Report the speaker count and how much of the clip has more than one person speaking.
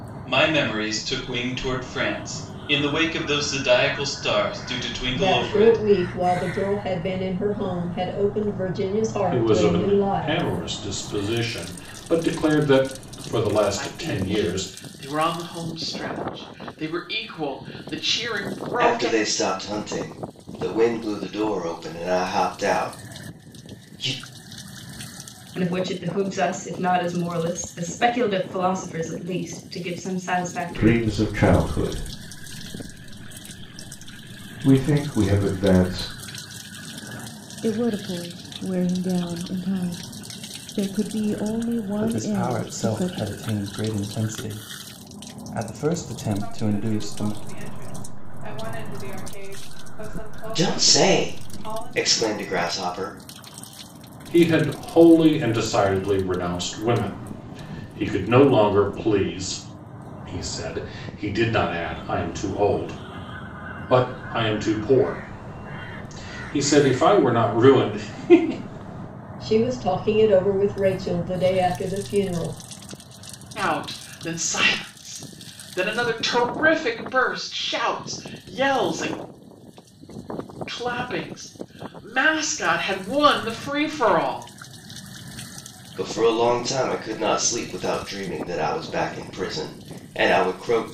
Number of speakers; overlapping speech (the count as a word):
ten, about 8%